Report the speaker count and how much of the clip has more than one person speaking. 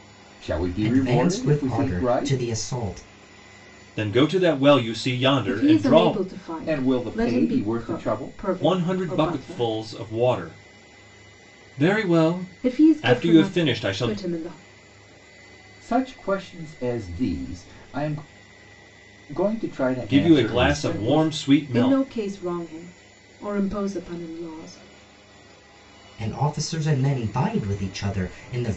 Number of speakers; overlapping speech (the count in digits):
4, about 31%